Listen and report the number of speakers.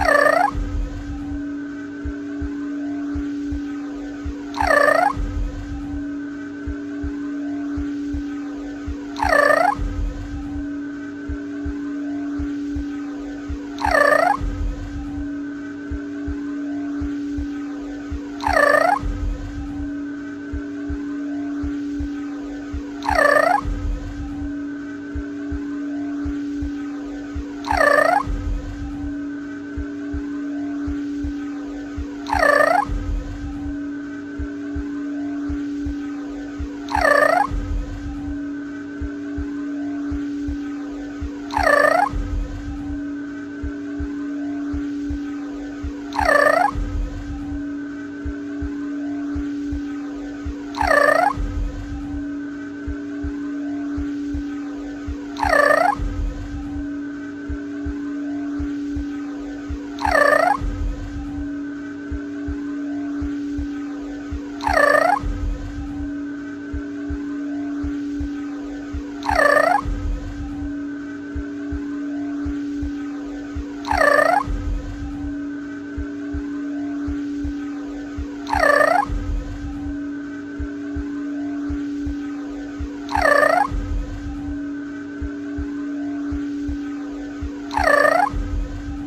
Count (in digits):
0